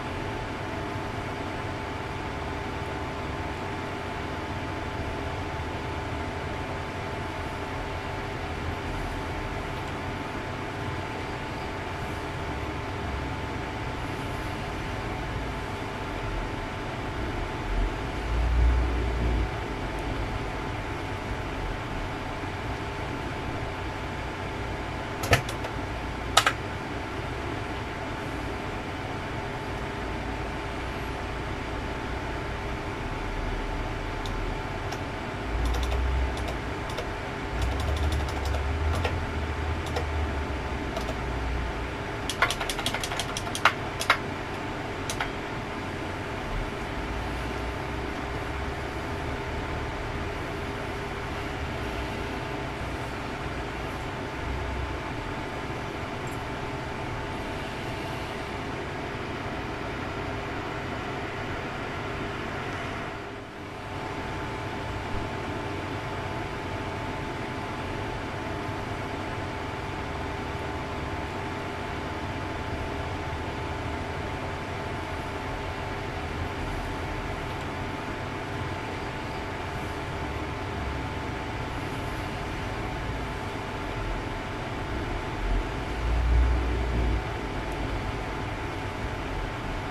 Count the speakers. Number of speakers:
0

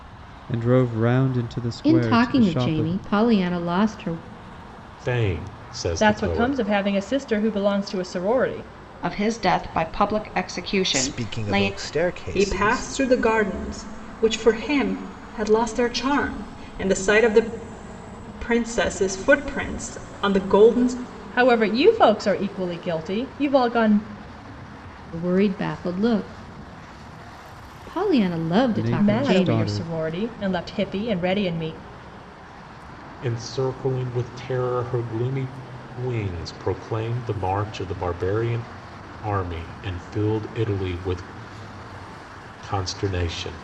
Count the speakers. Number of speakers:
7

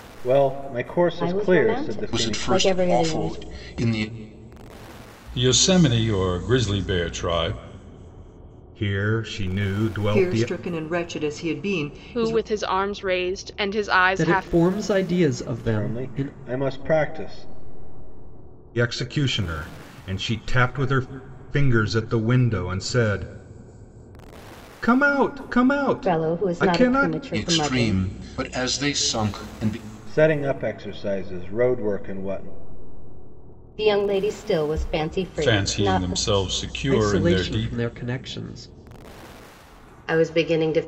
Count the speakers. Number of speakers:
8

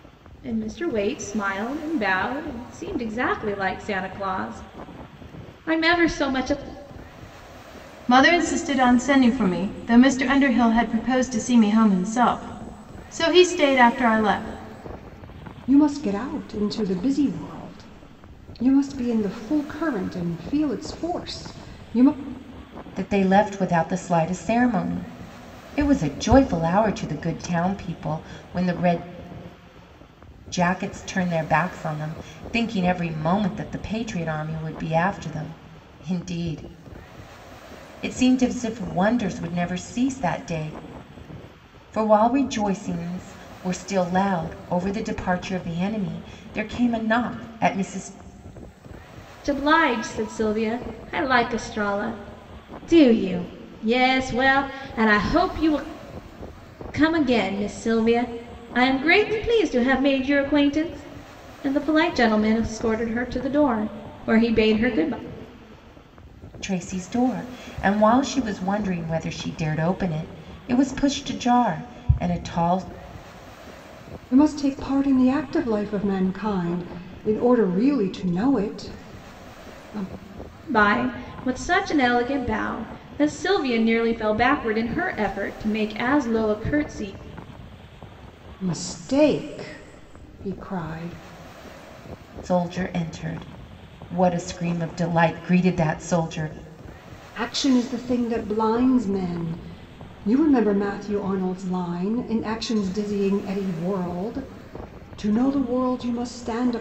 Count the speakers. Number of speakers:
4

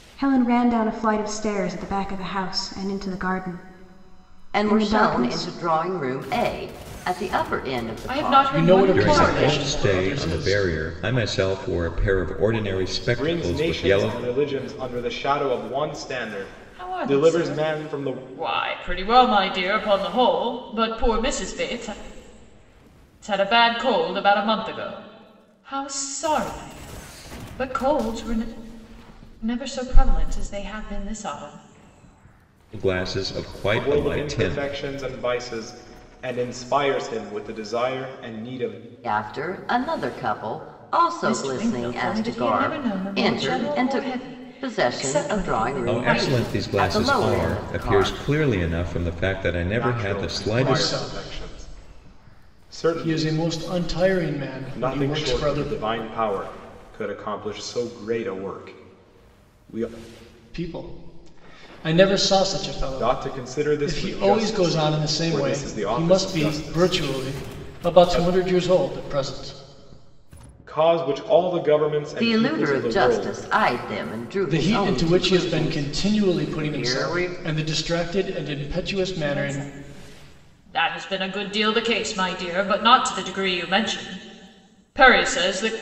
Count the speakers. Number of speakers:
6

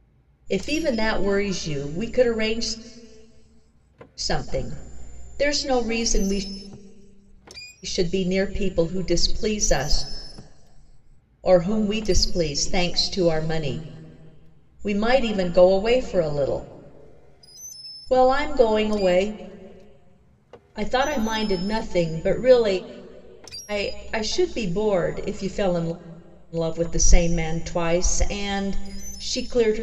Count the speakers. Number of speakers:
1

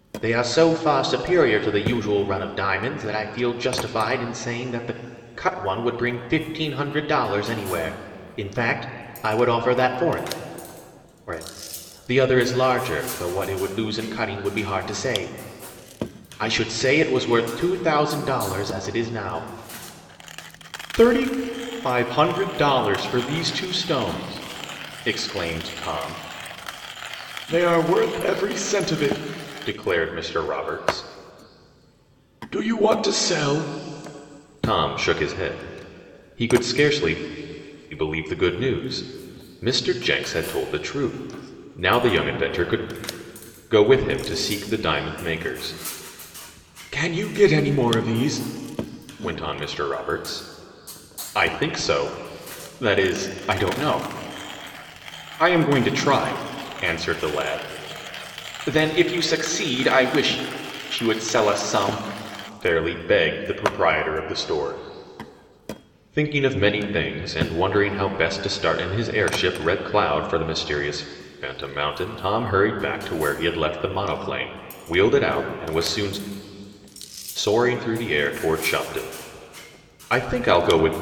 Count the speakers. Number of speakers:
1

